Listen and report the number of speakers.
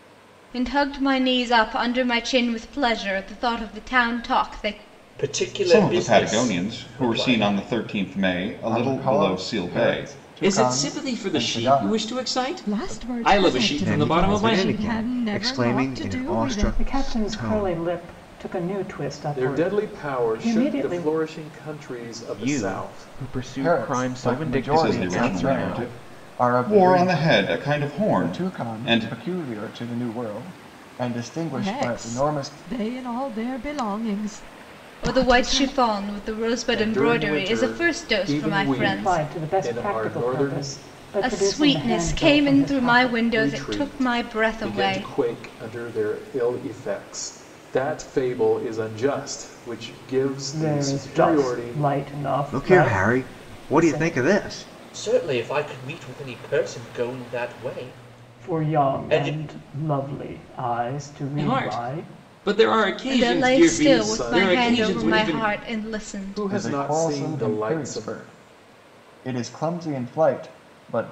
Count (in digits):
10